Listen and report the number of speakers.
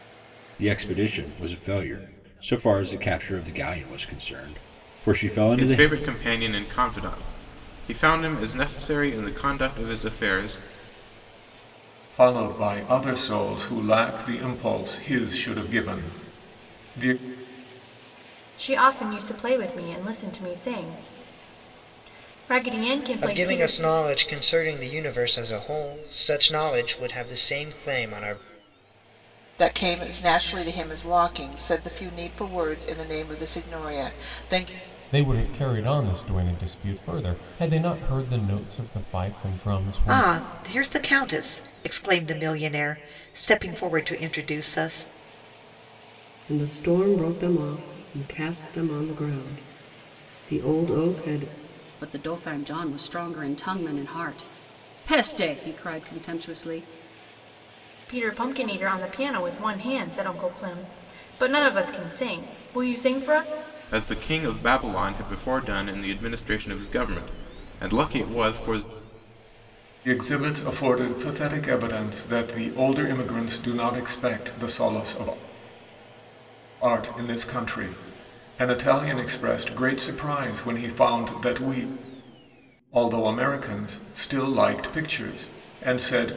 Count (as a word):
ten